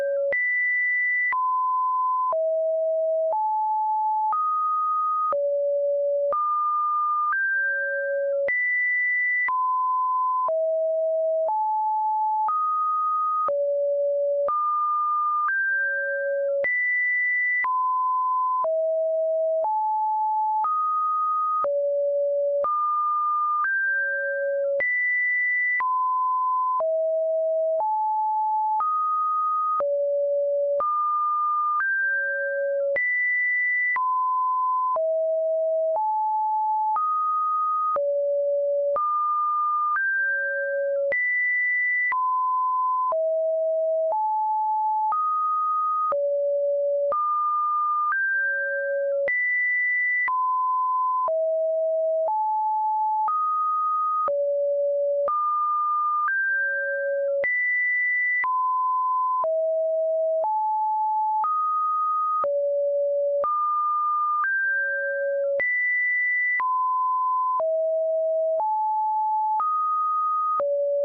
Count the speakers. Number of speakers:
zero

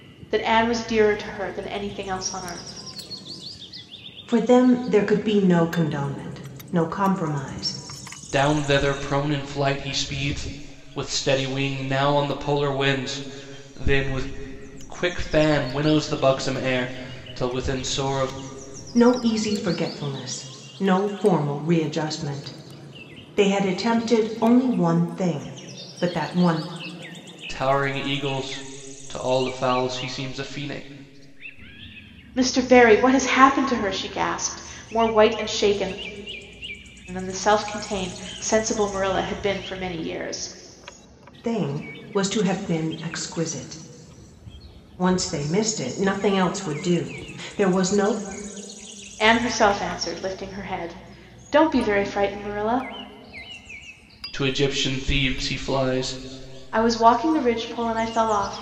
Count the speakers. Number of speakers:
three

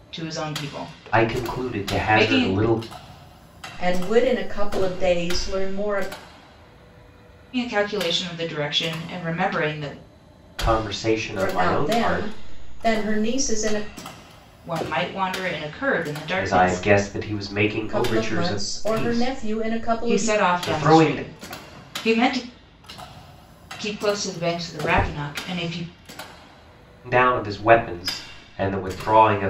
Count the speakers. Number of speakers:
three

